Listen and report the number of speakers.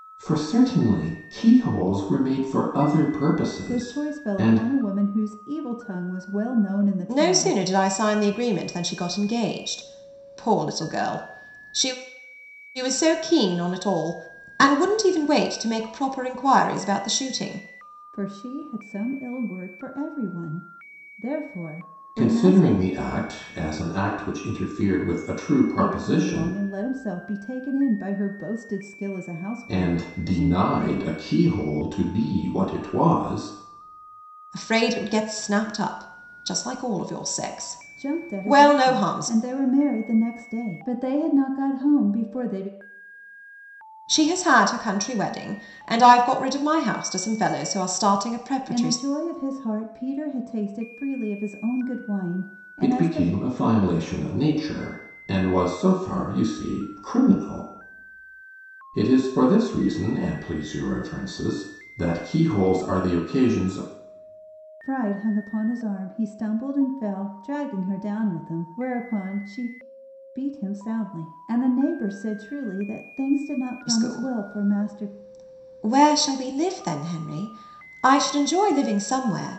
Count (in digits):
3